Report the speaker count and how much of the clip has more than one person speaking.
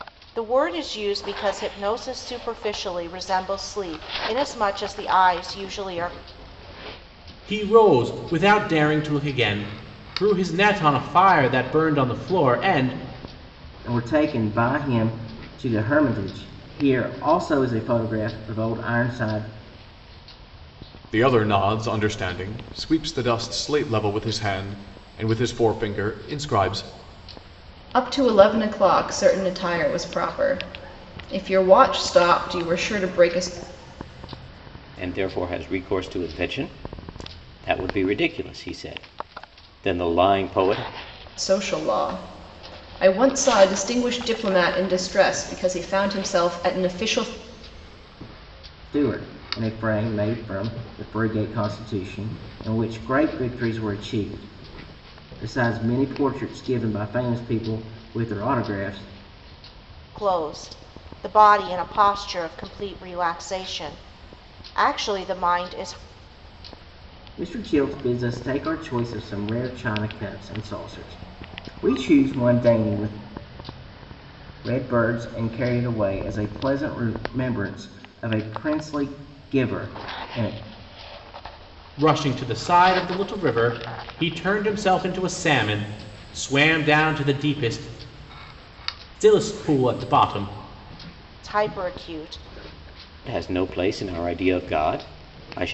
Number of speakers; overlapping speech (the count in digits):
6, no overlap